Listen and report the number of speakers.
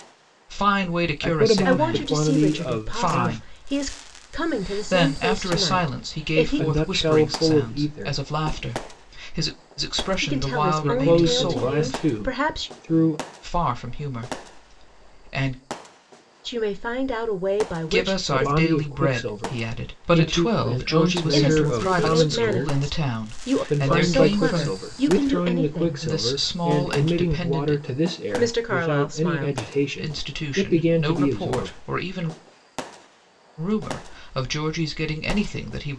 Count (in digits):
3